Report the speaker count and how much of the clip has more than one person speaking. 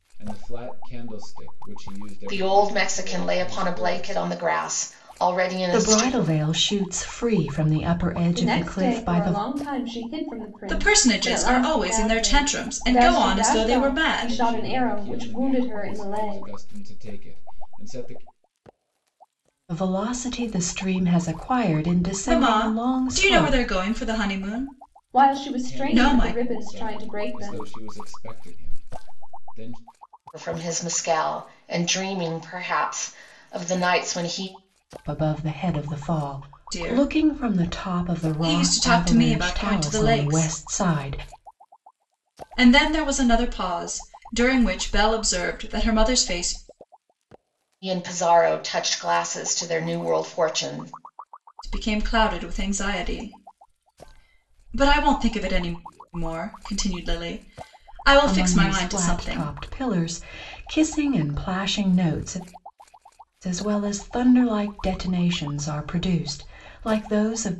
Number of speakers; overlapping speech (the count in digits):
5, about 28%